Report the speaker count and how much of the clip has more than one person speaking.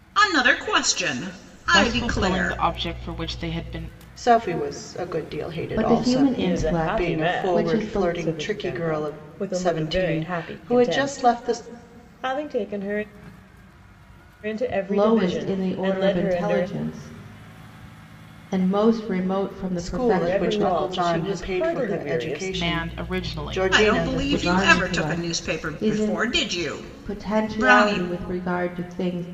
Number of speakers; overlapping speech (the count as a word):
five, about 54%